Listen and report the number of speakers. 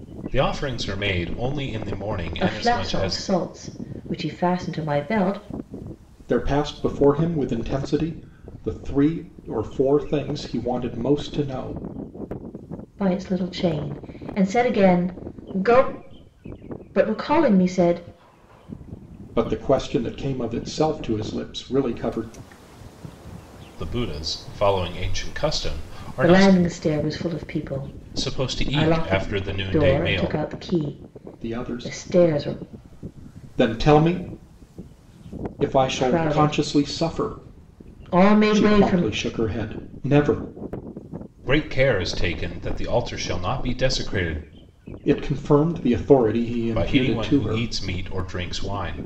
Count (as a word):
three